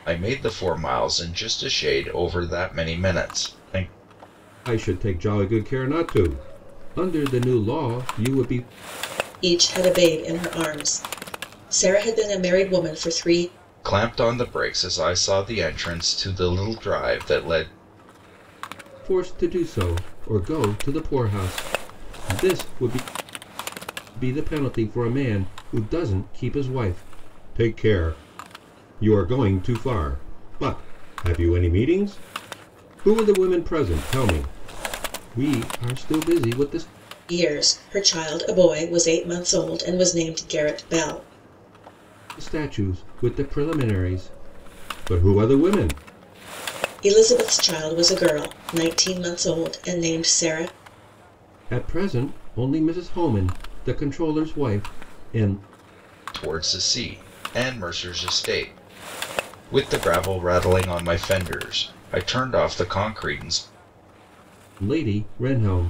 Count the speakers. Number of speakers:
three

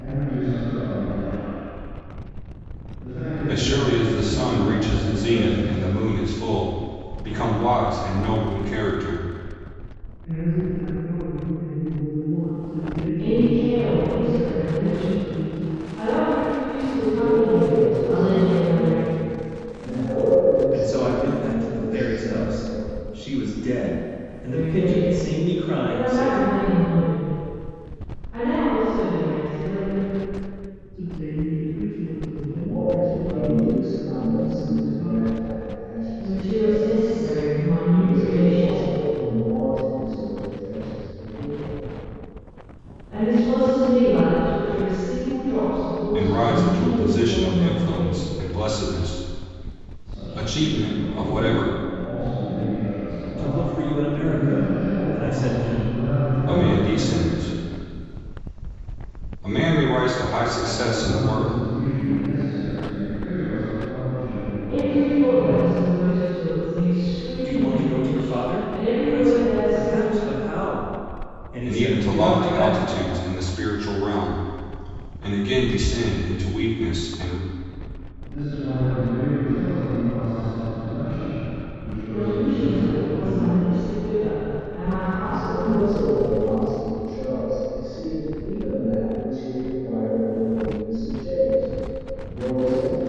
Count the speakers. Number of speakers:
six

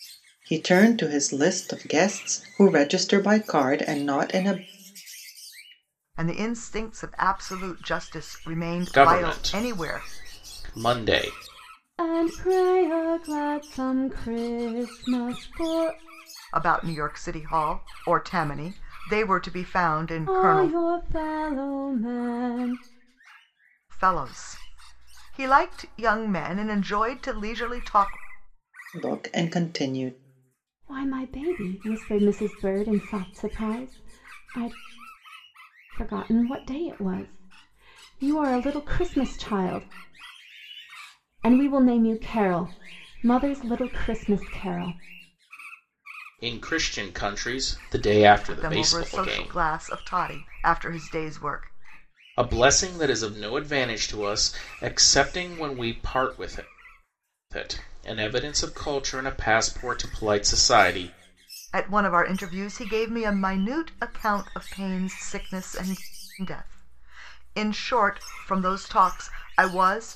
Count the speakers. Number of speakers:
four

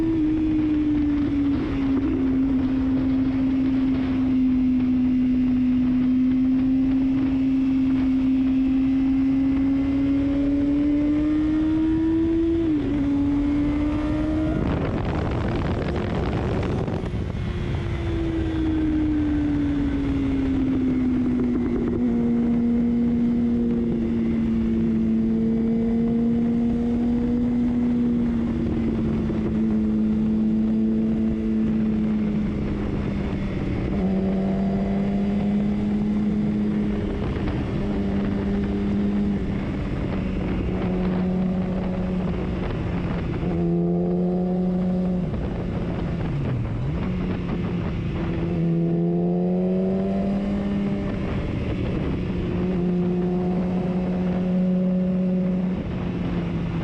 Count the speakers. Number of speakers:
zero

